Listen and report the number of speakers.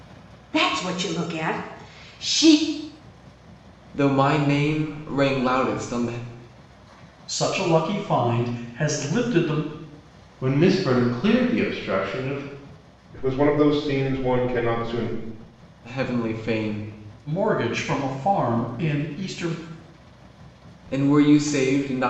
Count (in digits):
5